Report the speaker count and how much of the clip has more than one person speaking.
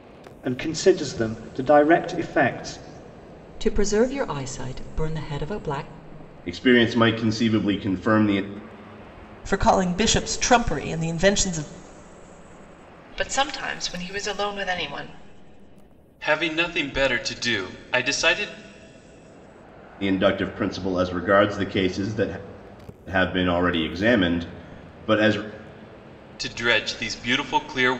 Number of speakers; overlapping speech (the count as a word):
six, no overlap